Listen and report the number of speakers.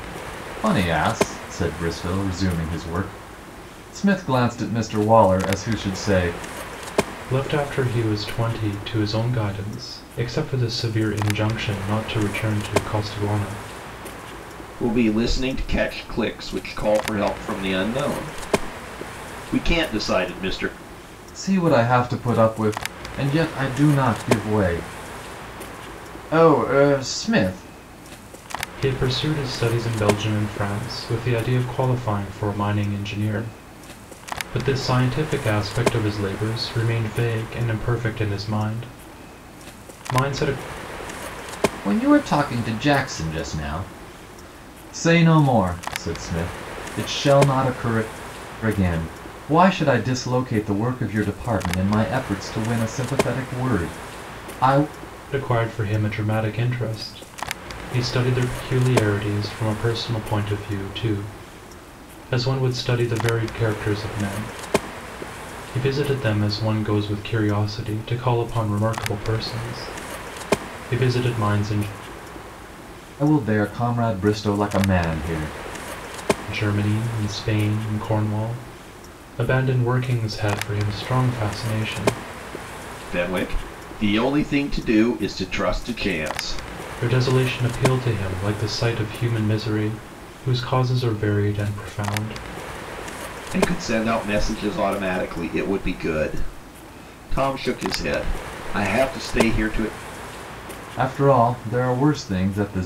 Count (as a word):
three